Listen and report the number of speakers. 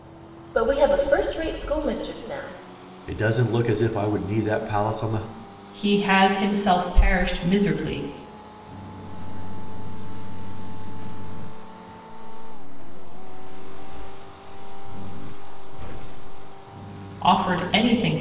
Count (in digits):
4